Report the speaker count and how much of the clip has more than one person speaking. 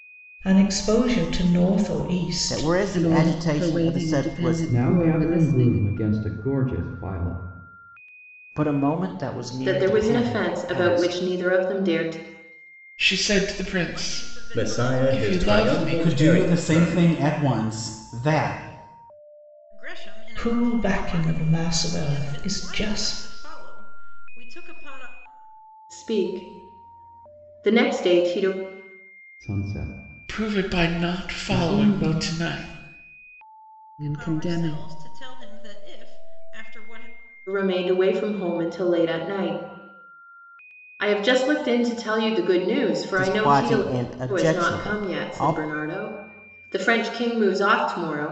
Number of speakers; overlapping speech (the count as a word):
ten, about 34%